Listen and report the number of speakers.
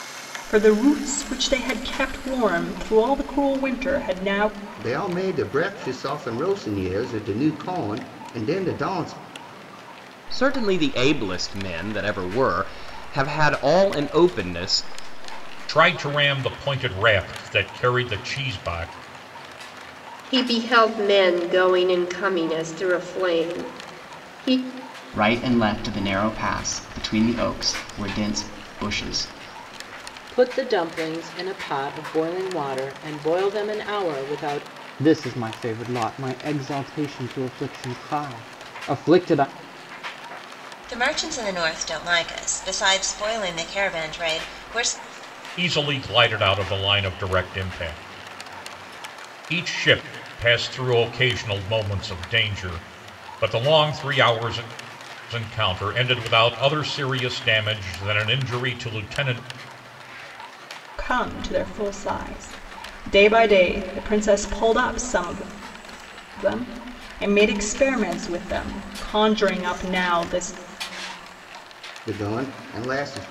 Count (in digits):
9